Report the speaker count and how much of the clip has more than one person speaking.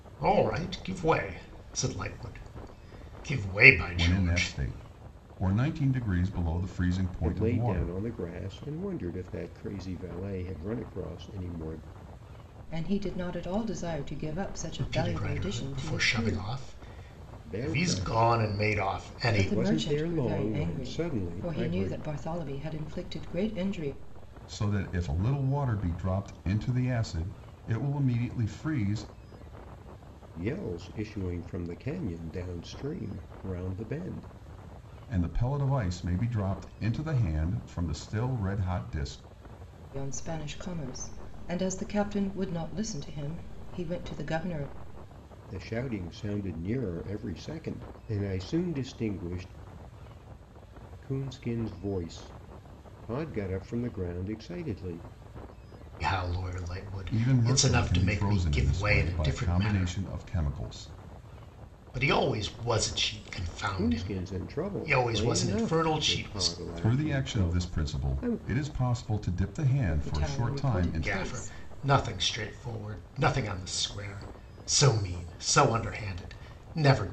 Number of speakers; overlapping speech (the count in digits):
4, about 22%